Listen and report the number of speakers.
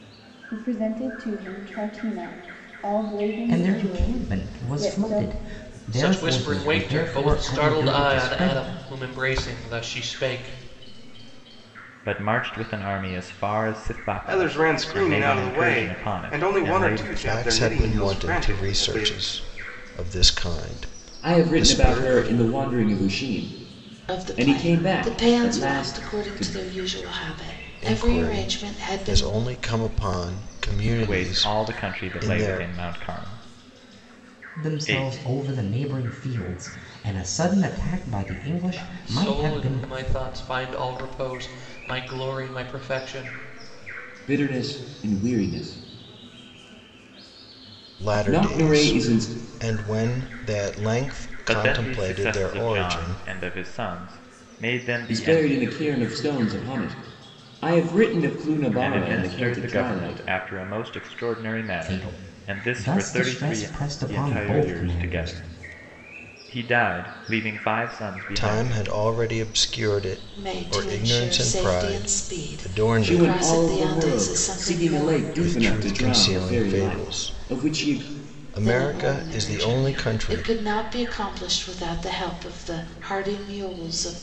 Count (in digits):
8